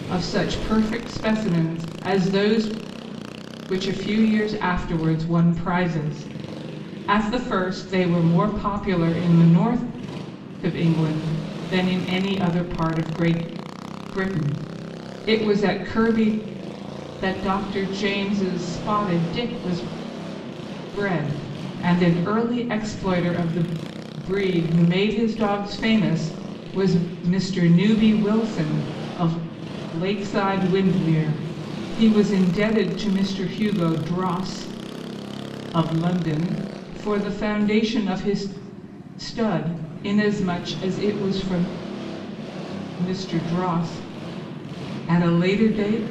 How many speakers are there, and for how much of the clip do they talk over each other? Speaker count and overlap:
1, no overlap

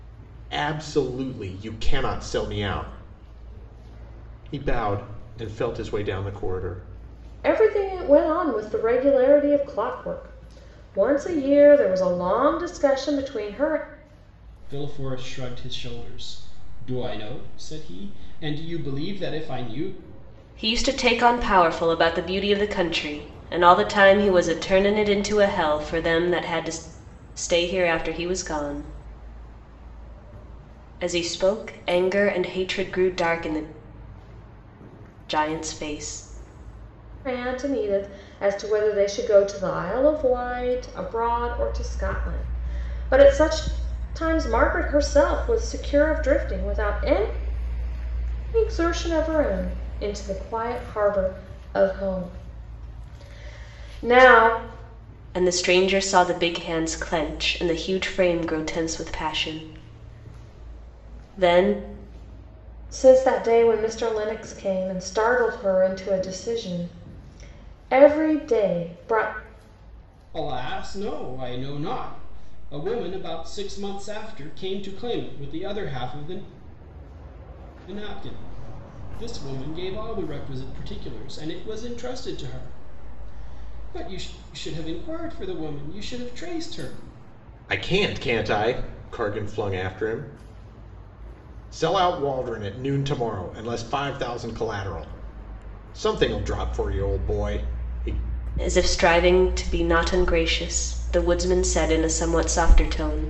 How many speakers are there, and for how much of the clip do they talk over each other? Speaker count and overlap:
4, no overlap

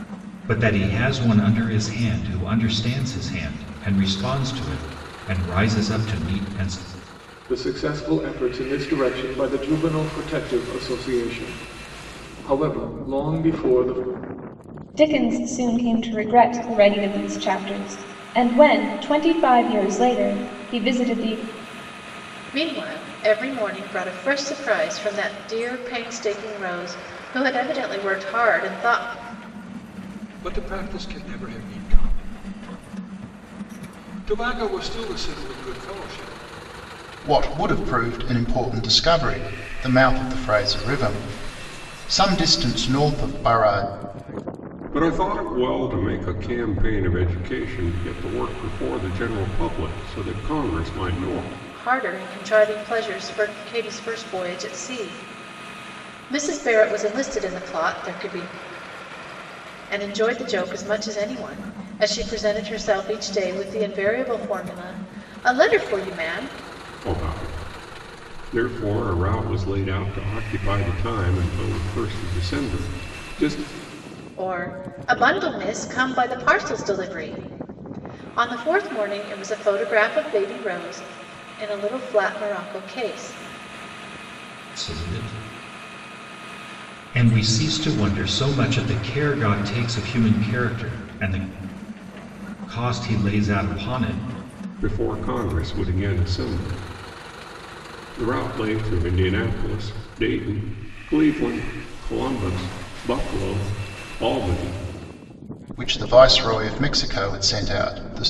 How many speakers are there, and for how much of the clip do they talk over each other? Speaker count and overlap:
7, no overlap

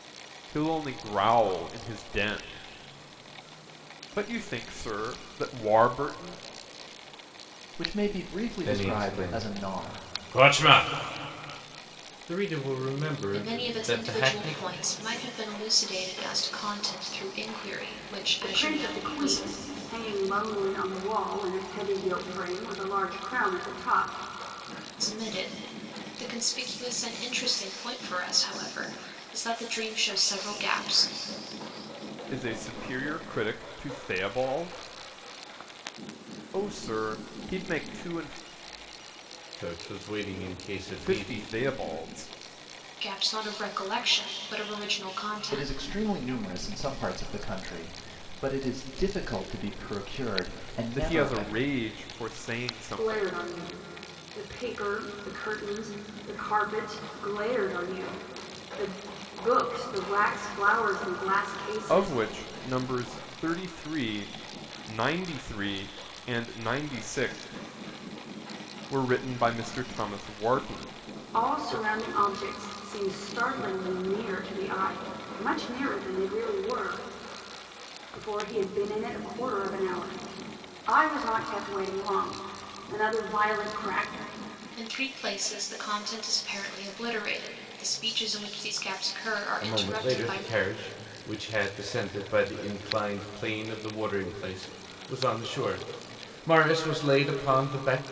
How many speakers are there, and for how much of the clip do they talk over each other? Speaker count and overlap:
5, about 7%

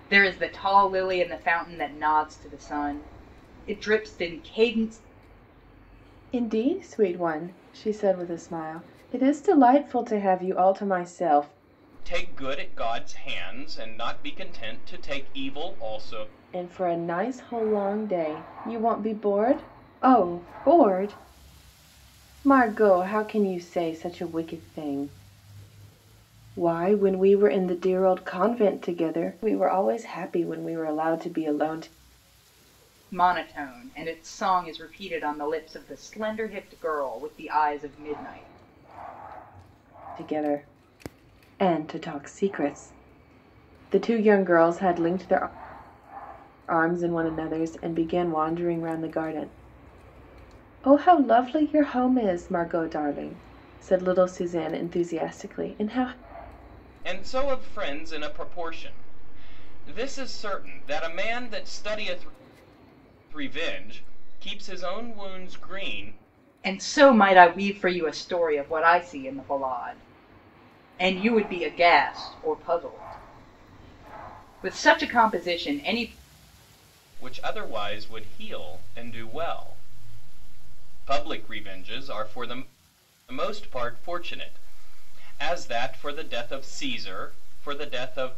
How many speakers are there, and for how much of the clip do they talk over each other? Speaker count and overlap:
3, no overlap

